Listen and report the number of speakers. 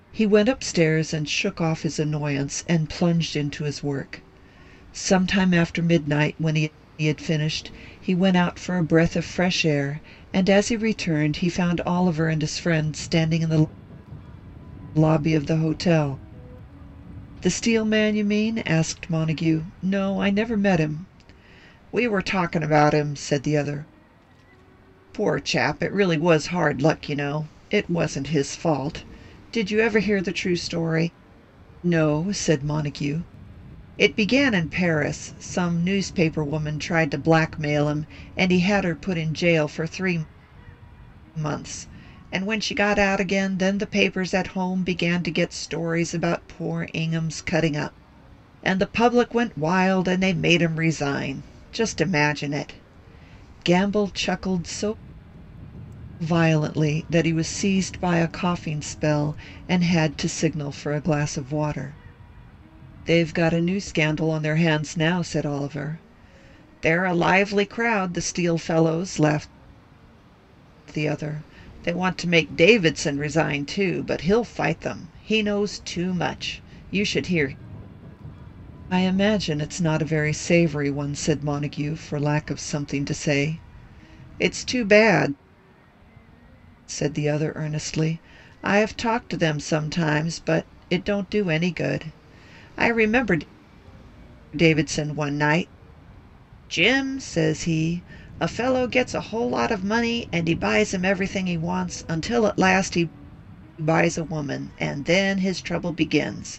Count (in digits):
1